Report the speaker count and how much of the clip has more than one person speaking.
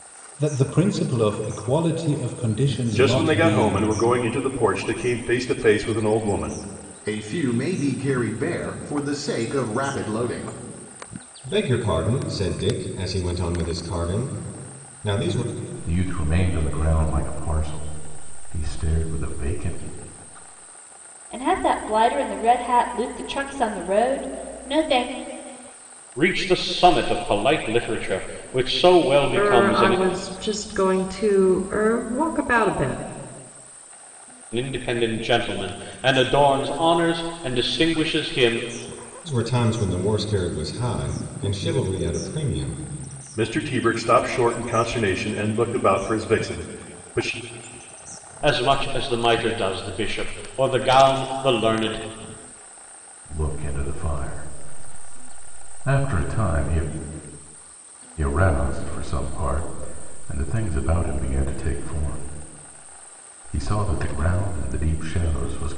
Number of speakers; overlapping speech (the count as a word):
eight, about 3%